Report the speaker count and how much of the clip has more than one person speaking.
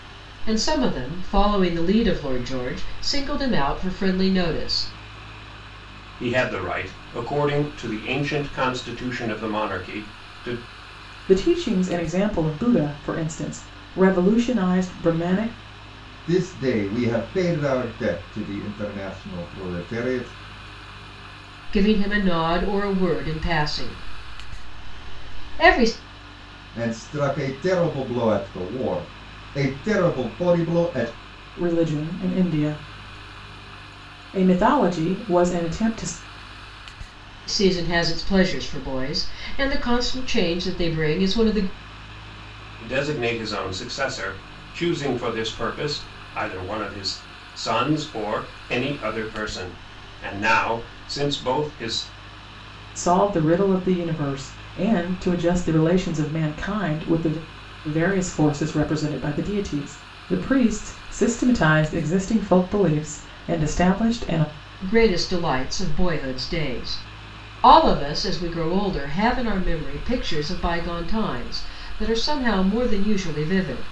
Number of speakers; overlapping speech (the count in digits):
4, no overlap